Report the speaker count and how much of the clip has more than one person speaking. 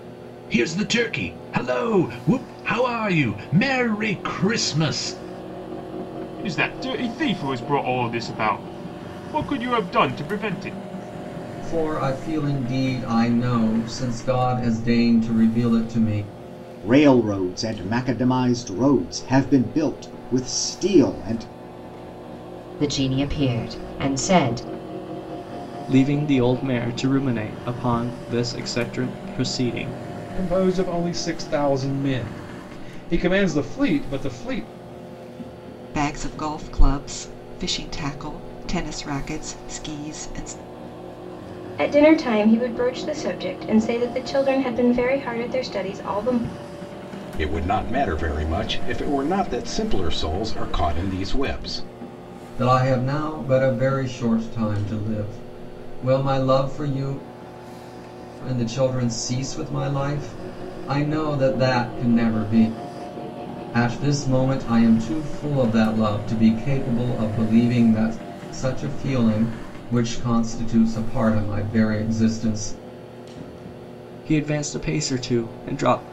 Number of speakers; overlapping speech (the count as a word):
ten, no overlap